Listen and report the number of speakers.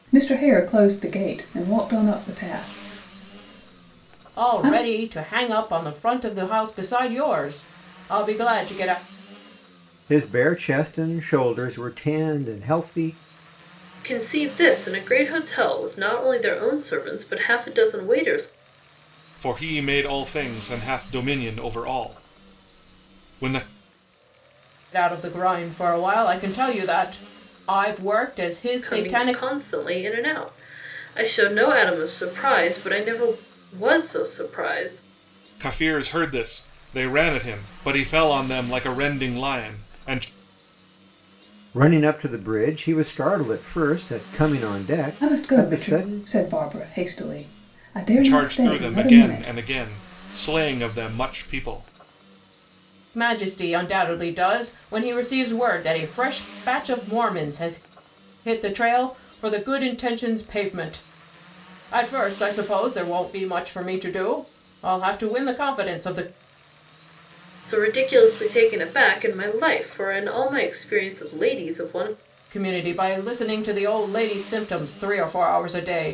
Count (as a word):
five